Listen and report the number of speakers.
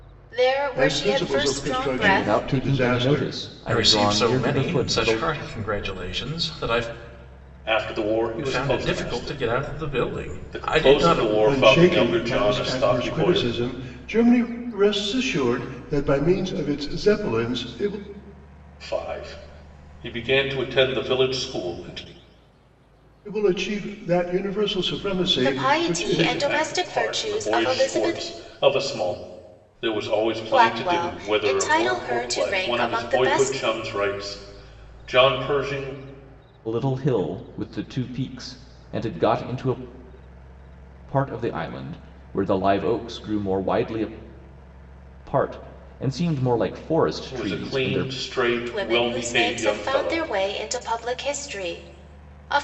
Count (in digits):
5